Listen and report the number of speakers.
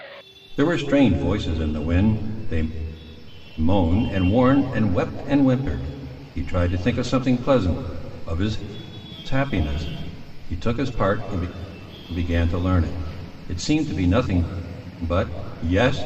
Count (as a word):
one